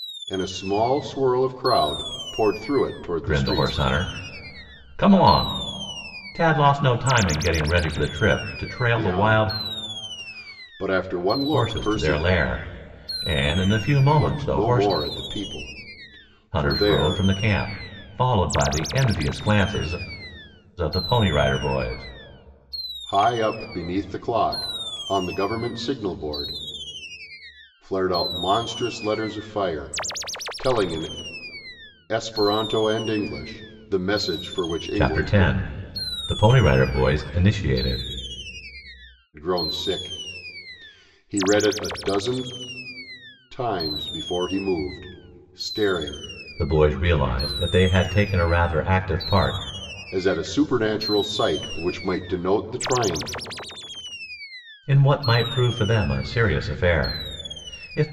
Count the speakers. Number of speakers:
2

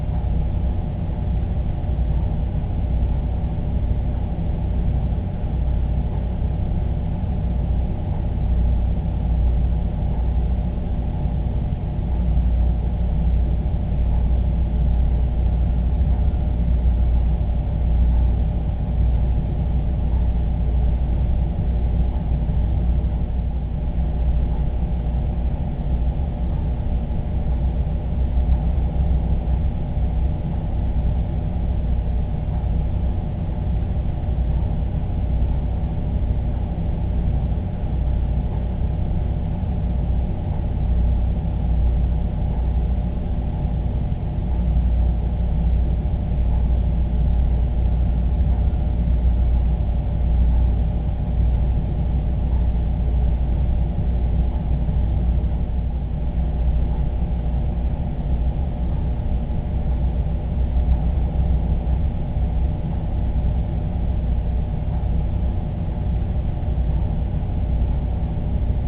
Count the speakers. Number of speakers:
0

